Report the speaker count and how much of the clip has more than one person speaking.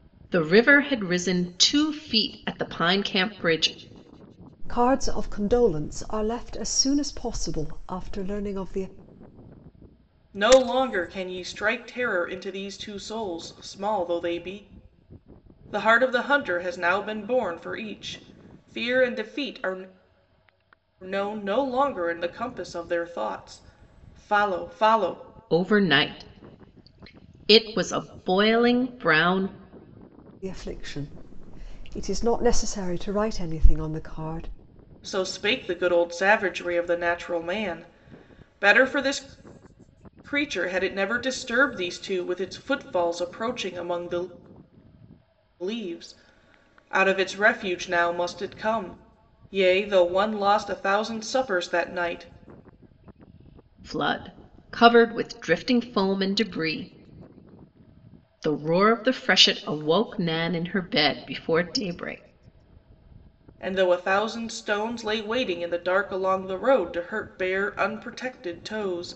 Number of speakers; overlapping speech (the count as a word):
three, no overlap